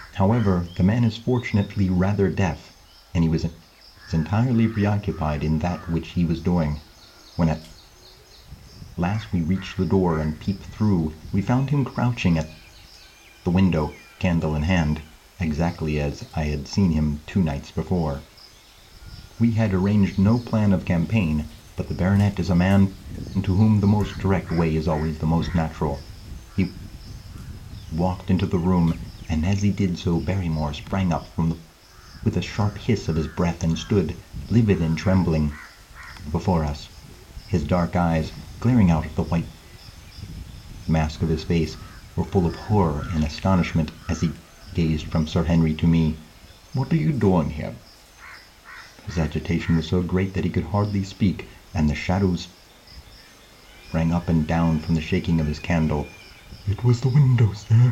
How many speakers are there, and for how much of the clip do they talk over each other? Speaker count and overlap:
one, no overlap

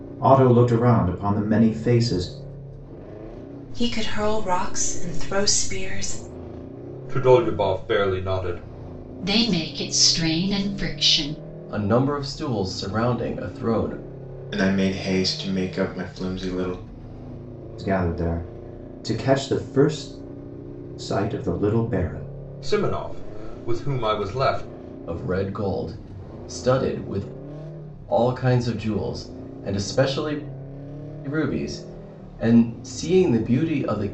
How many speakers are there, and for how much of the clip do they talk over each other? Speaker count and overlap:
six, no overlap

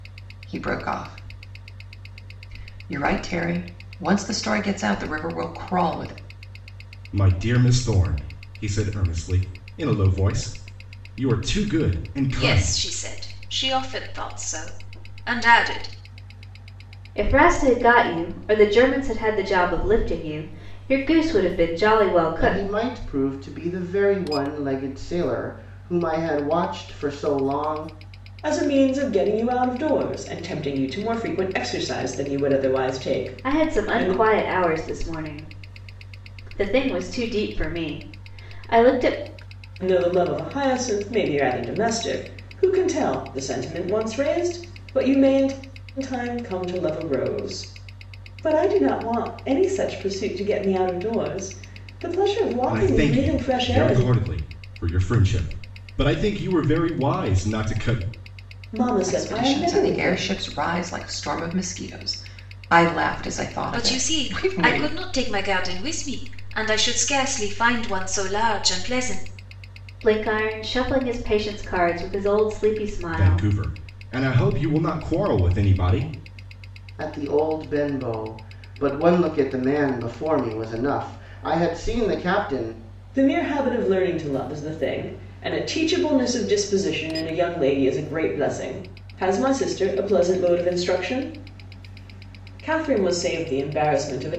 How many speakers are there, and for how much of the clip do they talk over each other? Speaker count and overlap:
six, about 6%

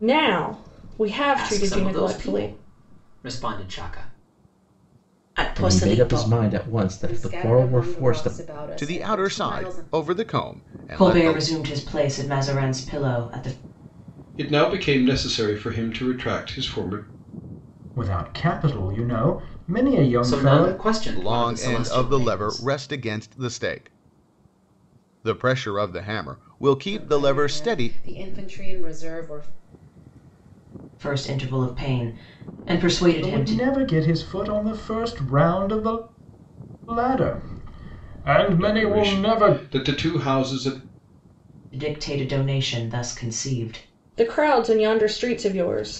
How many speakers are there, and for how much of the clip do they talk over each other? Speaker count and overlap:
nine, about 21%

